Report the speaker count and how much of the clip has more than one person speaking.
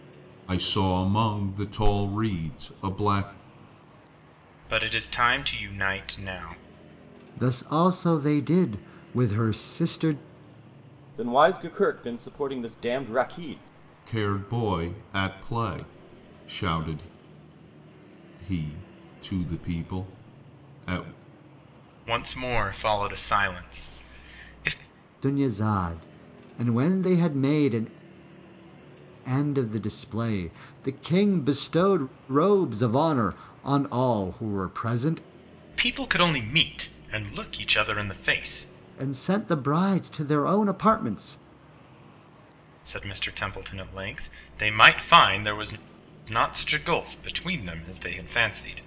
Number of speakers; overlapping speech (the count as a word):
four, no overlap